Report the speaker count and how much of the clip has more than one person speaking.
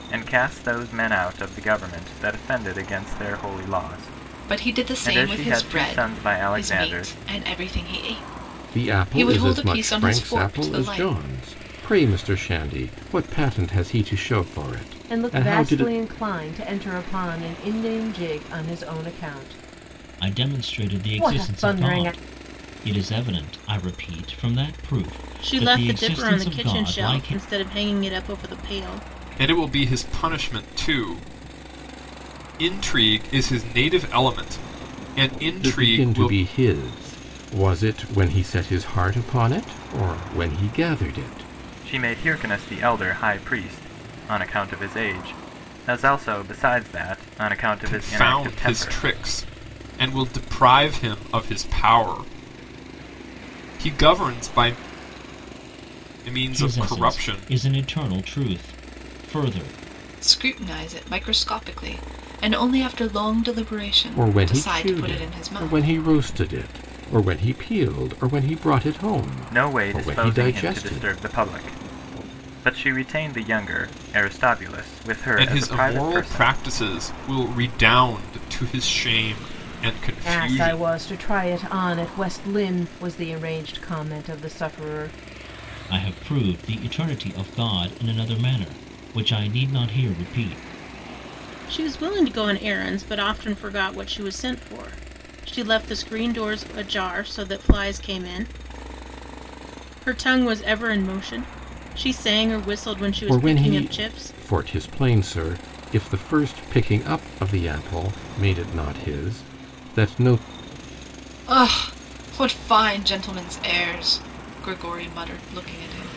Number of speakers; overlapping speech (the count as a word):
seven, about 17%